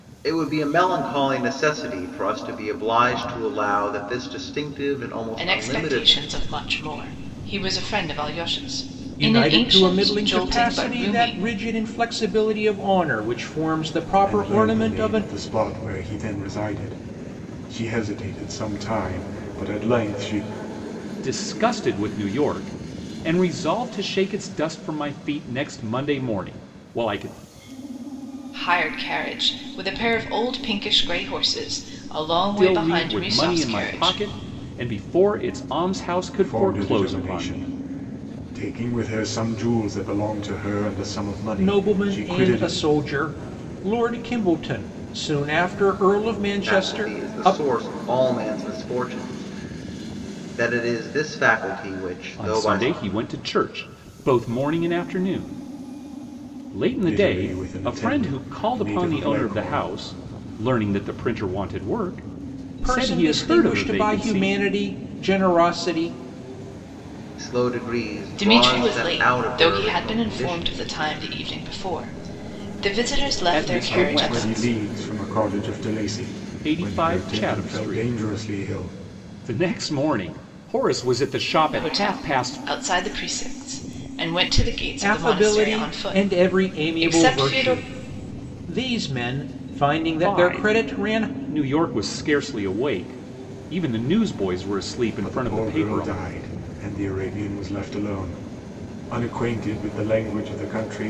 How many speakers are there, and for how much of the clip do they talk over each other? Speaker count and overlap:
5, about 26%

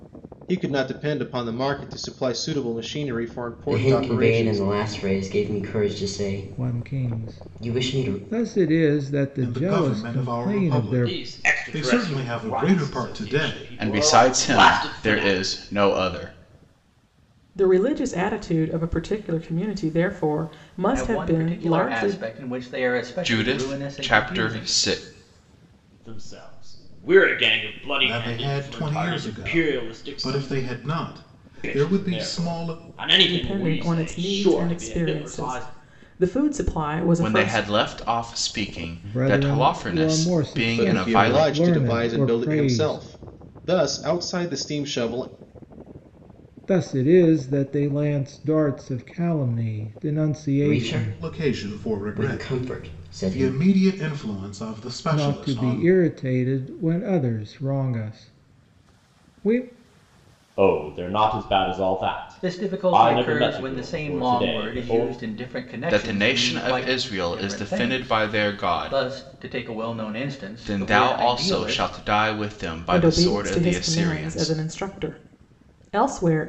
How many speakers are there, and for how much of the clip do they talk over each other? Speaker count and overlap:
8, about 46%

